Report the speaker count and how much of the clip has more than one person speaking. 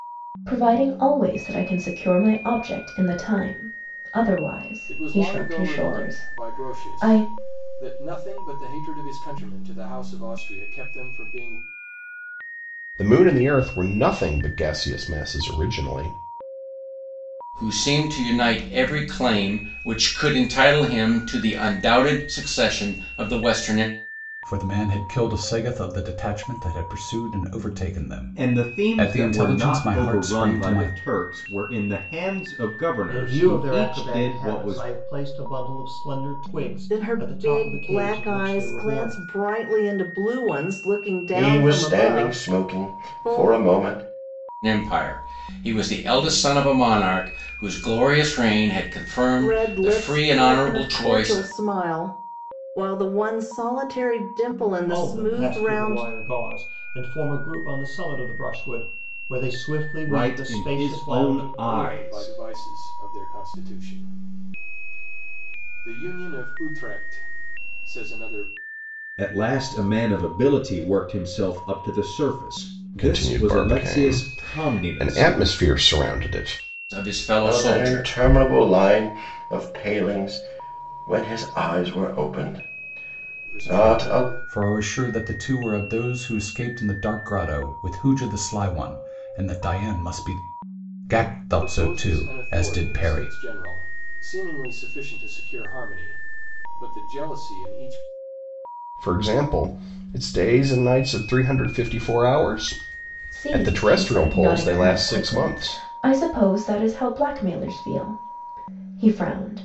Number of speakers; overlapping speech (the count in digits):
9, about 23%